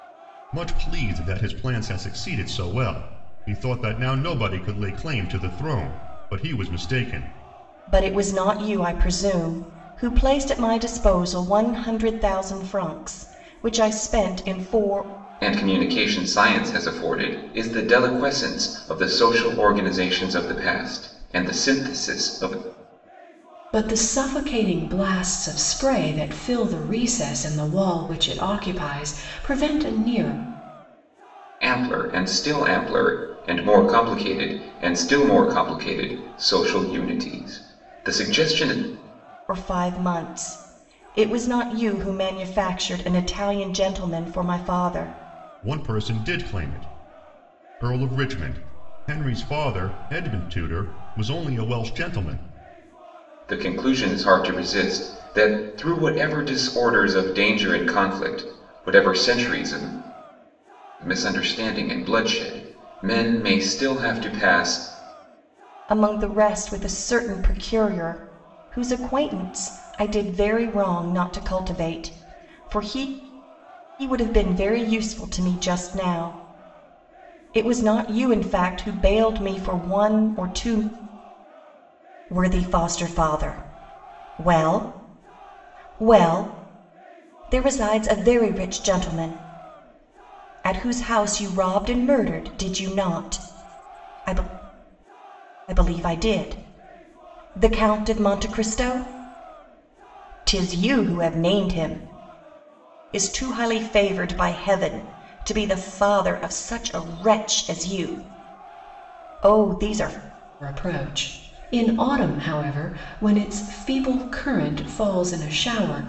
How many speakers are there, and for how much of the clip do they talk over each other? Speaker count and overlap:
4, no overlap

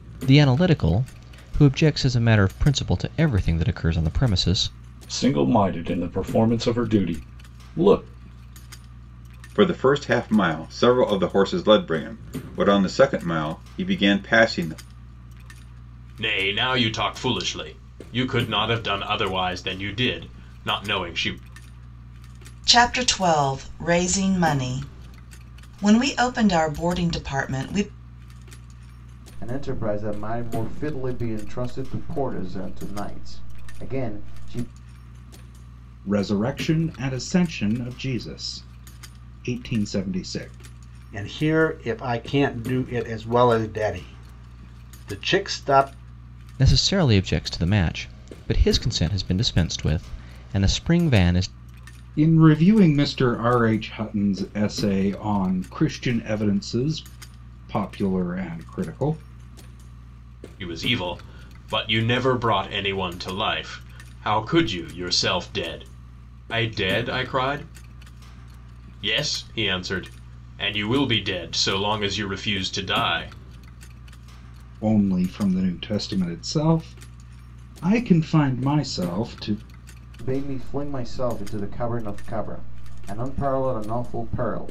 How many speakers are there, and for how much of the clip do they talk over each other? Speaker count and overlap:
8, no overlap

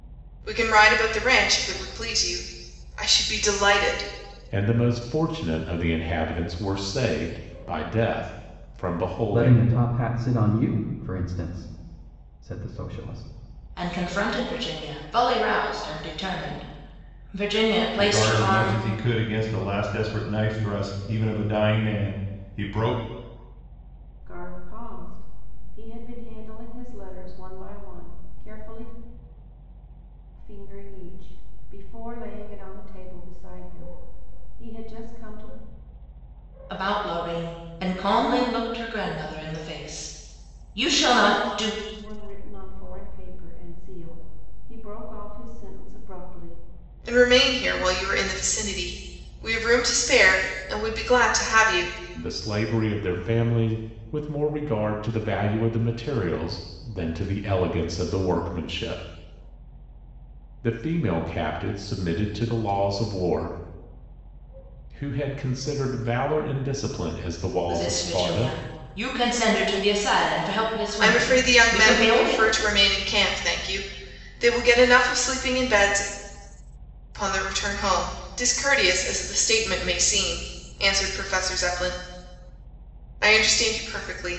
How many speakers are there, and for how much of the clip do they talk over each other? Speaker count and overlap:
6, about 4%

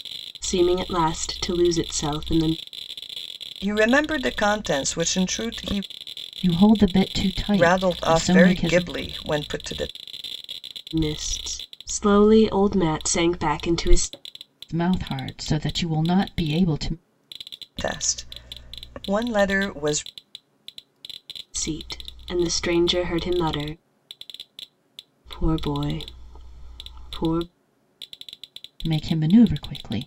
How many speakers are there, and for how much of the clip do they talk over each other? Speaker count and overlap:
3, about 4%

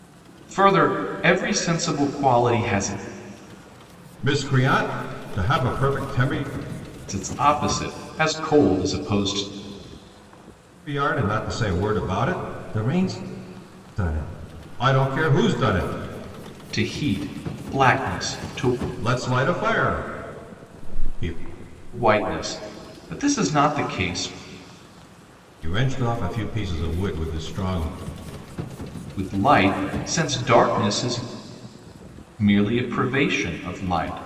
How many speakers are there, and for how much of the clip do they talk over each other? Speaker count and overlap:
2, no overlap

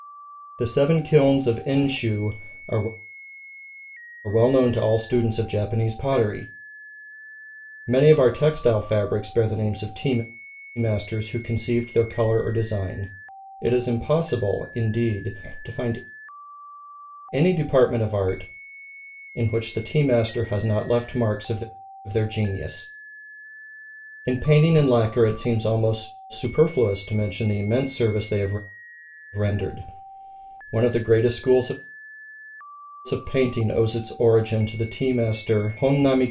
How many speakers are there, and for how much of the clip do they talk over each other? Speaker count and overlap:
1, no overlap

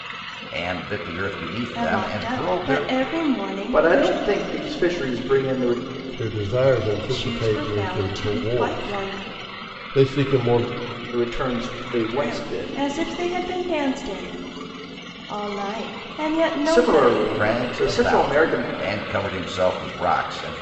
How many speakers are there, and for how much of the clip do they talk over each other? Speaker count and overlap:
4, about 32%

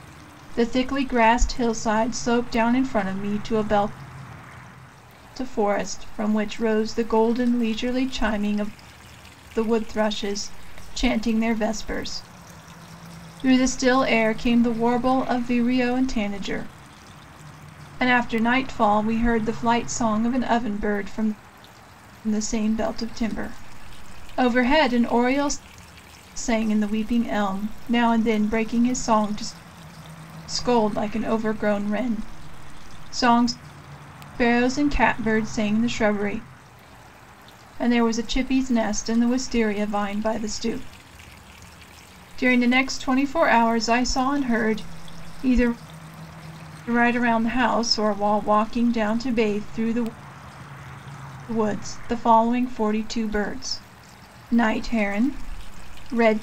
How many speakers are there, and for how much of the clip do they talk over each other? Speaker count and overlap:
1, no overlap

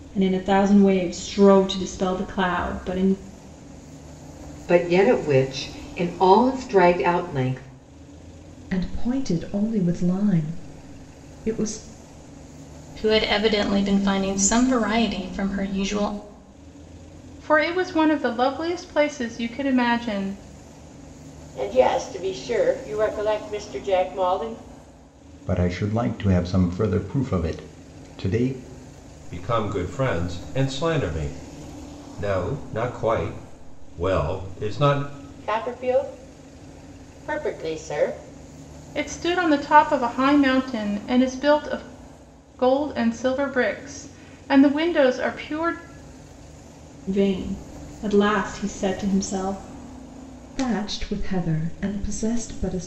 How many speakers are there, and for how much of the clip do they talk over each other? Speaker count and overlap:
8, no overlap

